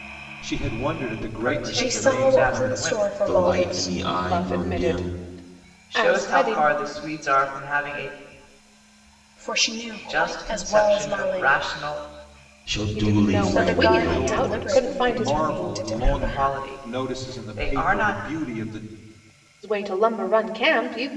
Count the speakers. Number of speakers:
five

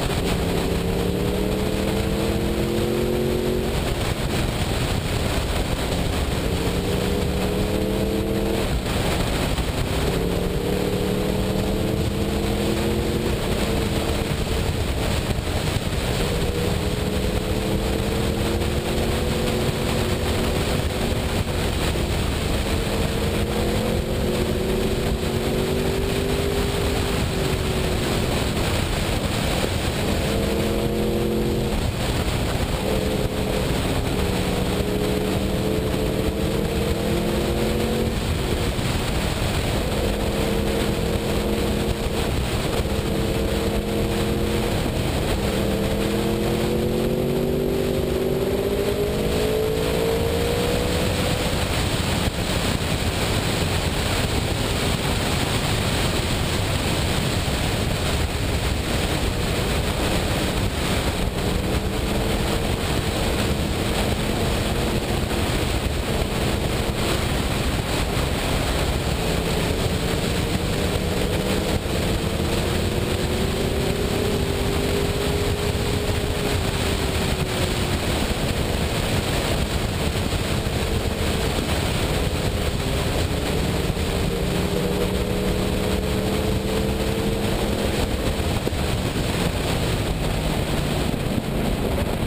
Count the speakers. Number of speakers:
zero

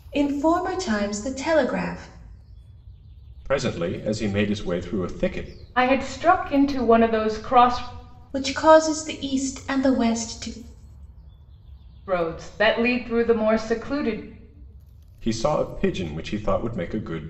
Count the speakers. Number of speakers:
three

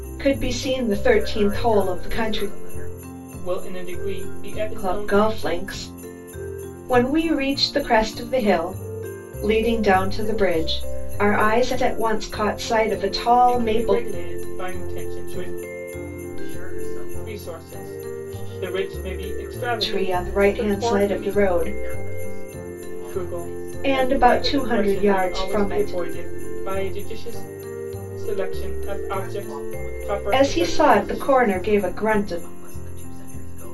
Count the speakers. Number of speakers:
three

